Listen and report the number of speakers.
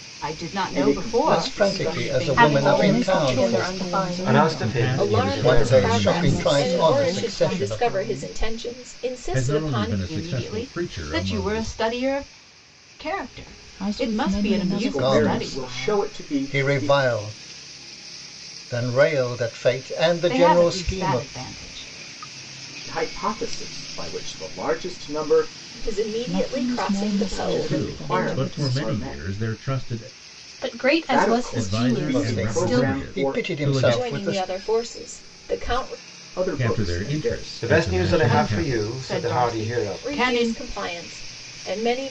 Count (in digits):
8